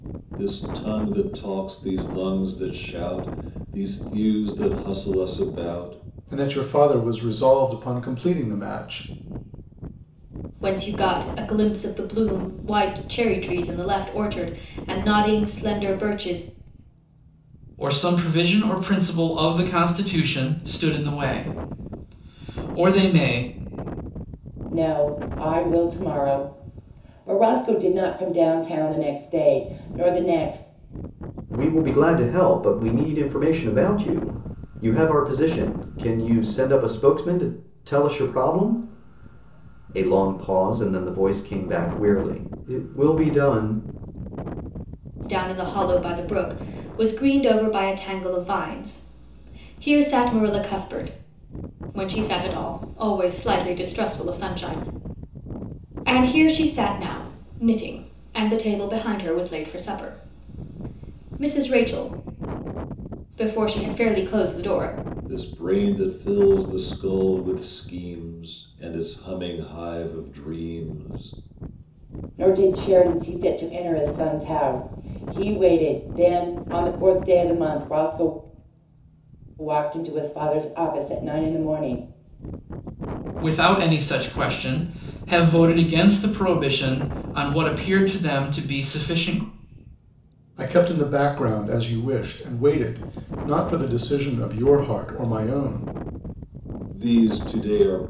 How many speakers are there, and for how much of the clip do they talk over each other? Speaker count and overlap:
6, no overlap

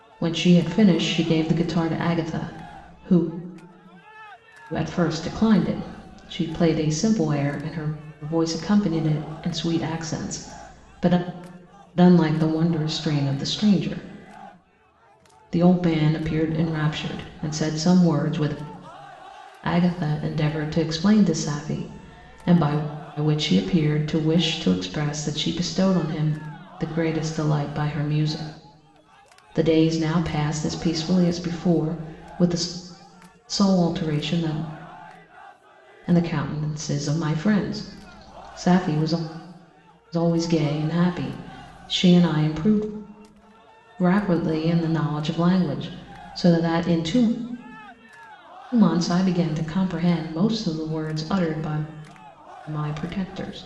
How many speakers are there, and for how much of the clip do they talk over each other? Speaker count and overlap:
1, no overlap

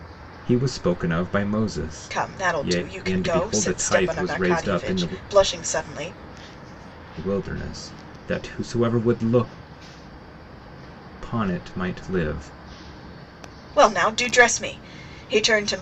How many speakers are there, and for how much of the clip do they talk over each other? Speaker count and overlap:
2, about 19%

